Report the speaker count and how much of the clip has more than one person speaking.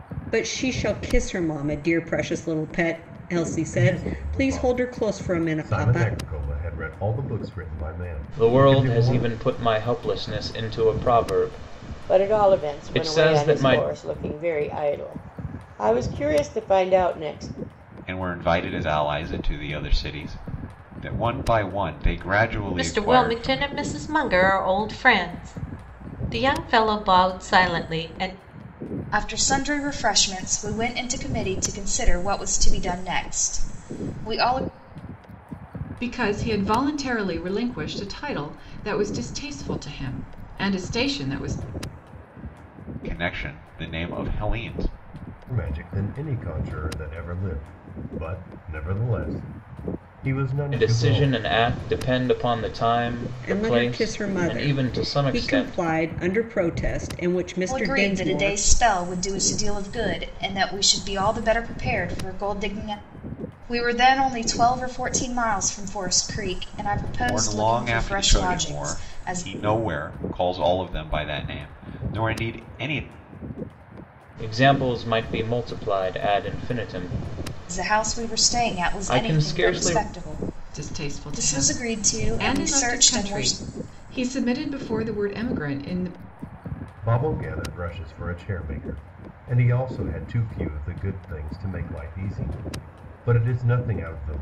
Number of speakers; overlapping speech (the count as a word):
eight, about 19%